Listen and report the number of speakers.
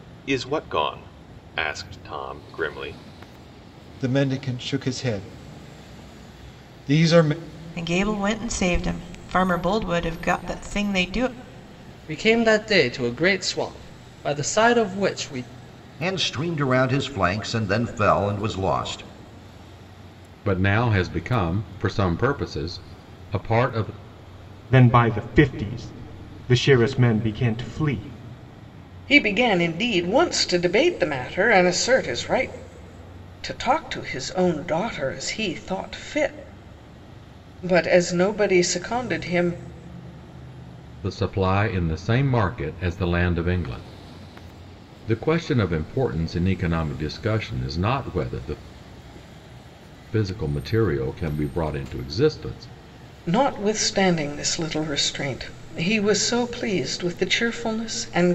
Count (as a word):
eight